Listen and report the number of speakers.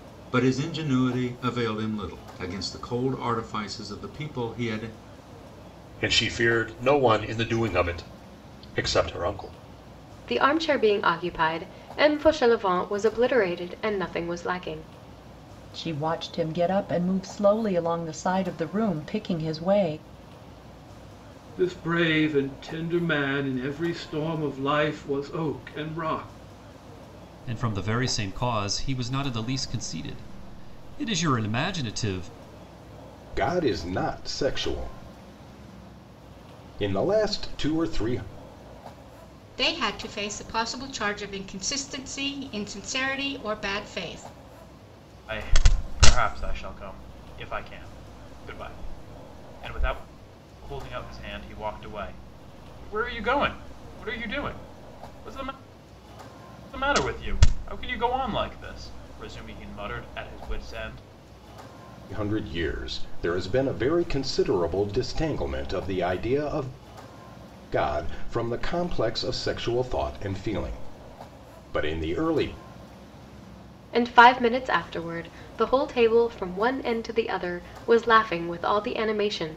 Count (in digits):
9